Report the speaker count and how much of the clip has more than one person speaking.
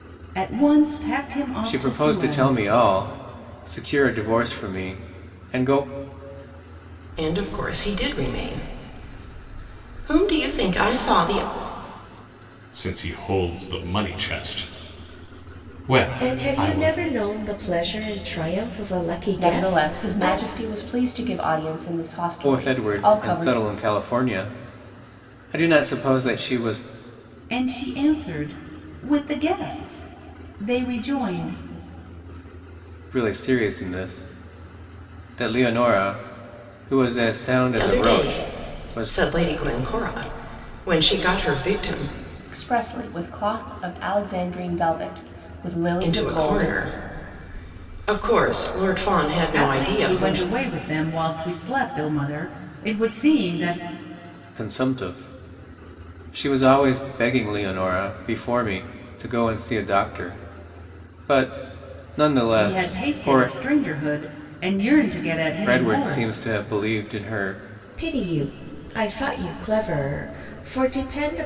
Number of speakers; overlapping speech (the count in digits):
6, about 13%